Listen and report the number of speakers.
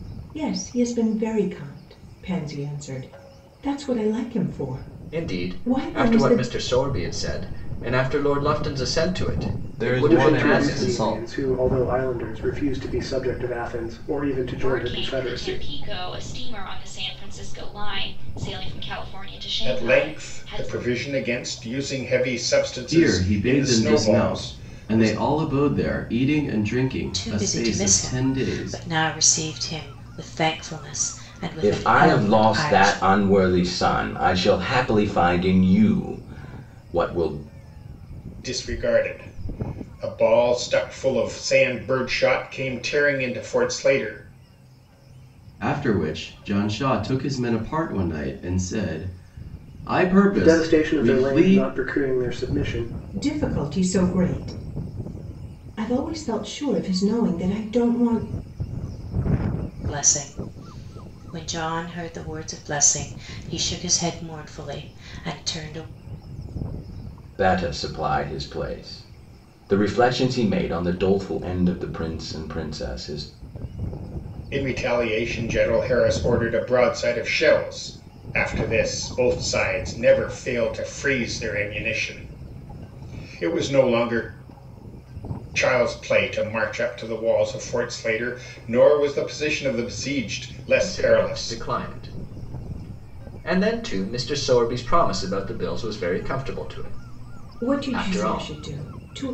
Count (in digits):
9